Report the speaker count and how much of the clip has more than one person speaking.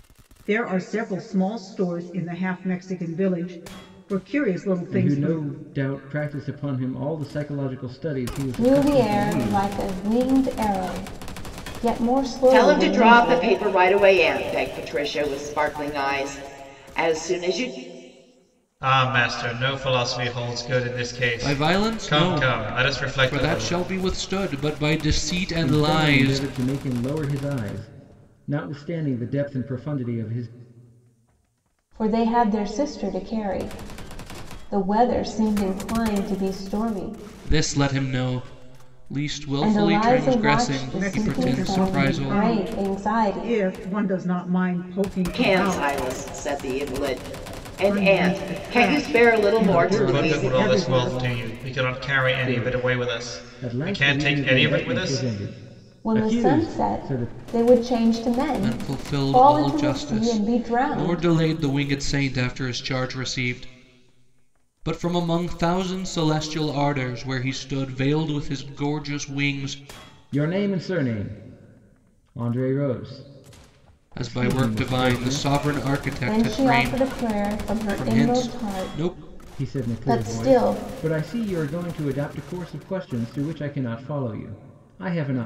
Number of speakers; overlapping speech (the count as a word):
six, about 32%